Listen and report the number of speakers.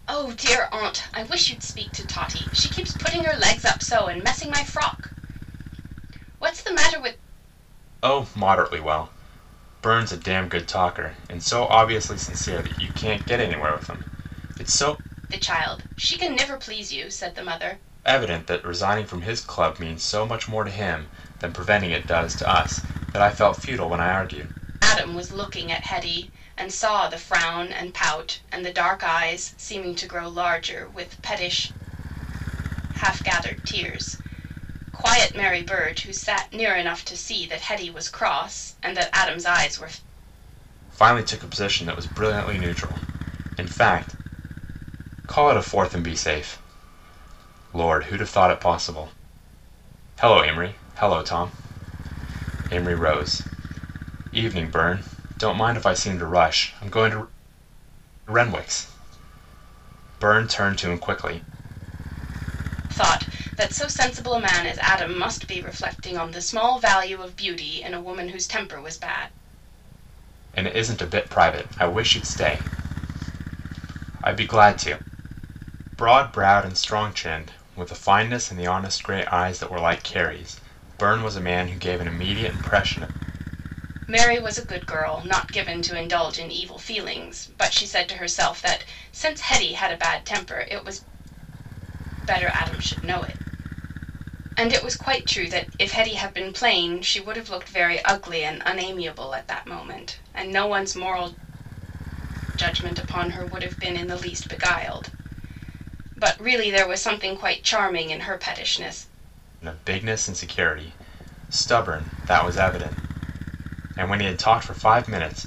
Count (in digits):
2